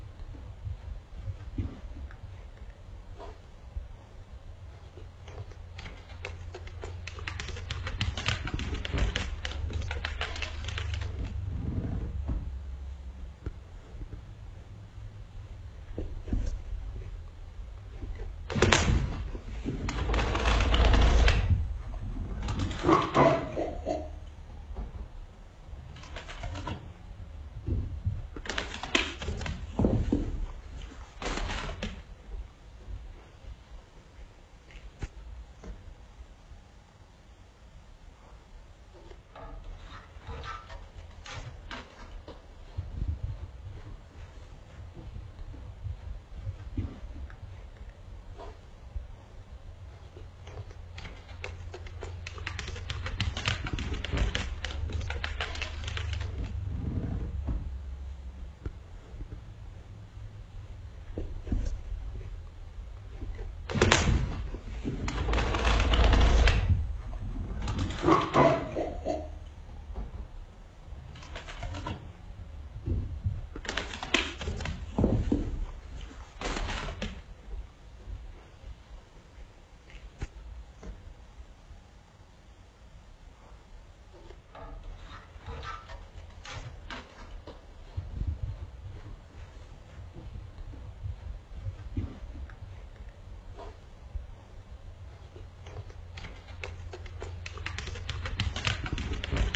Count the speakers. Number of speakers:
0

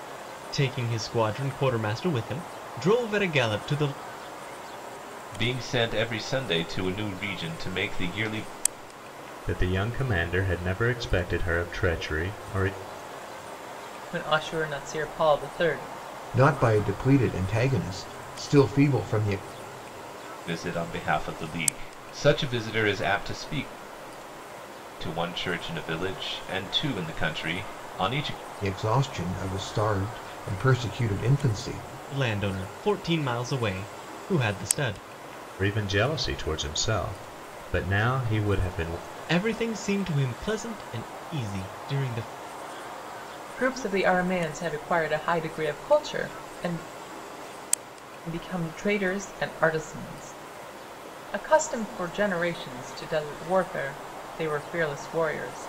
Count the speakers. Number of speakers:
5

